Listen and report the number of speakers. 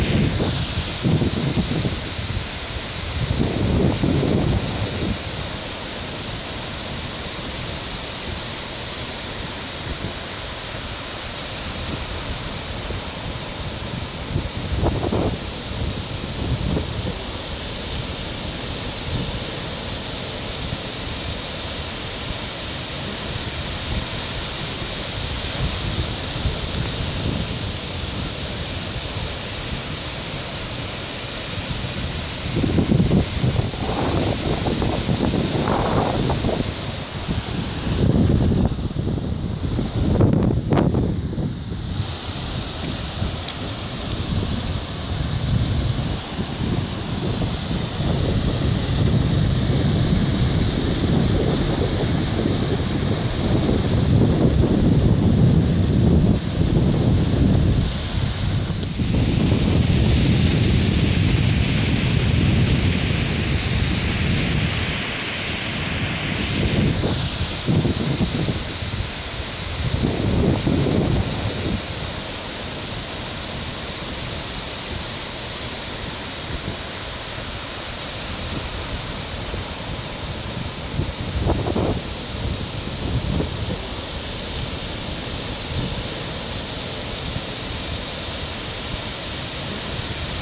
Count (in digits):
0